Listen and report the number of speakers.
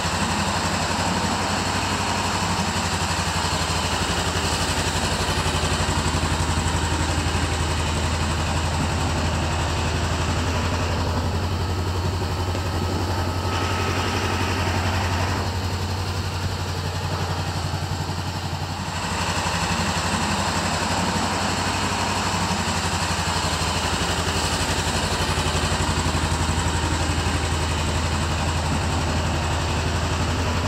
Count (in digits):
0